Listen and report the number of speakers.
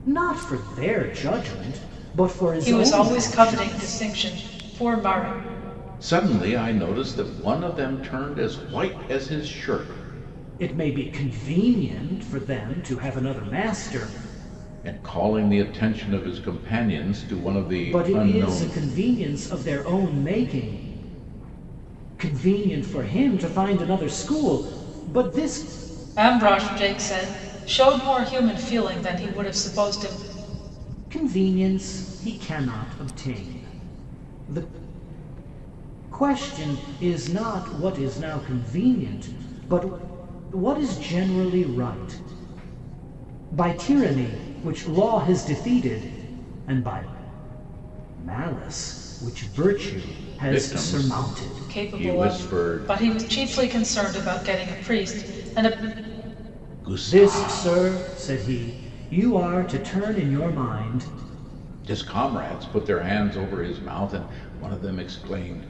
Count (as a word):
three